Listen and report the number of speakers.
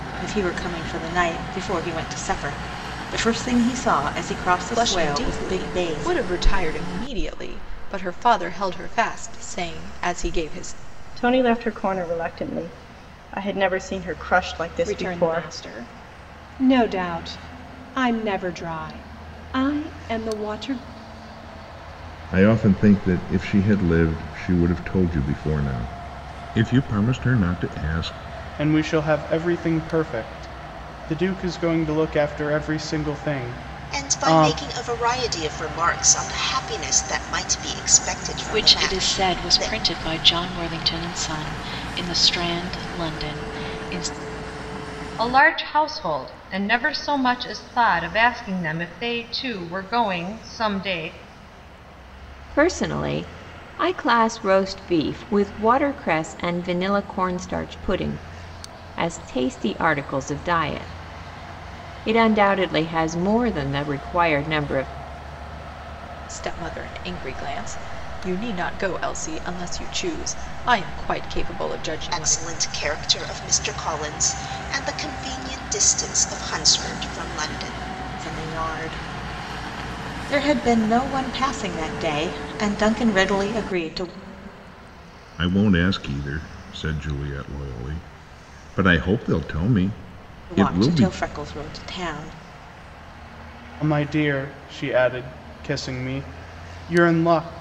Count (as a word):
ten